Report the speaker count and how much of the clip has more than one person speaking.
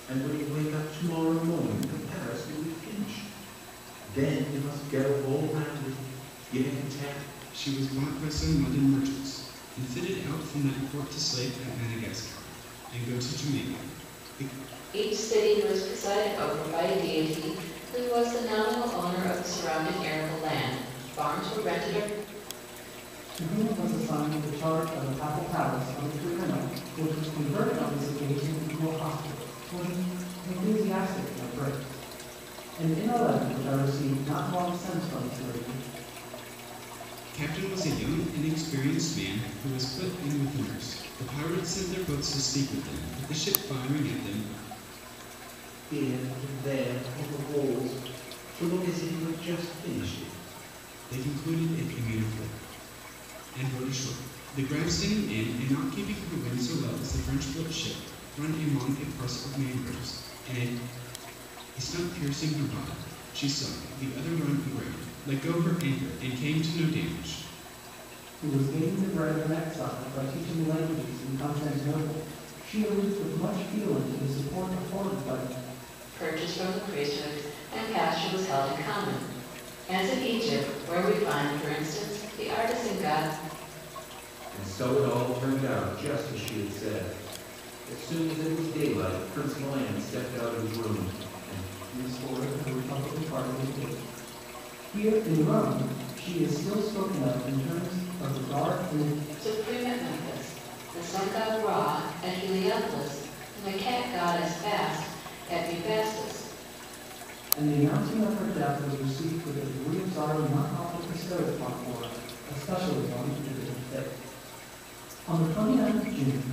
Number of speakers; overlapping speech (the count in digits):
4, no overlap